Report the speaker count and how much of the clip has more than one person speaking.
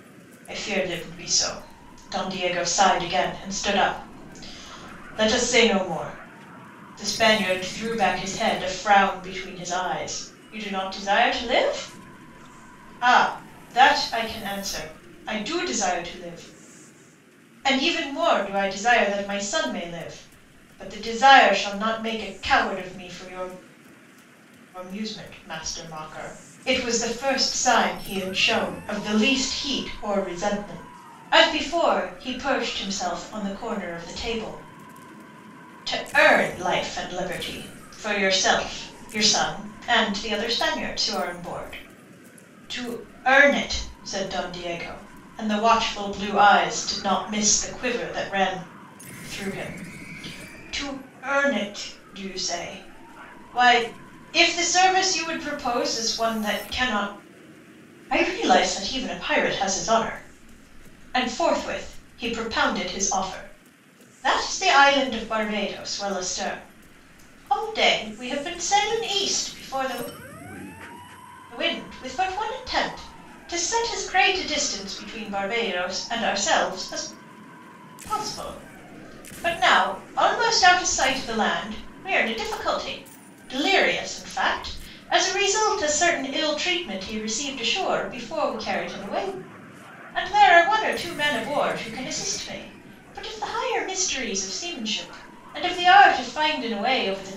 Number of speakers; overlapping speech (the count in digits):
1, no overlap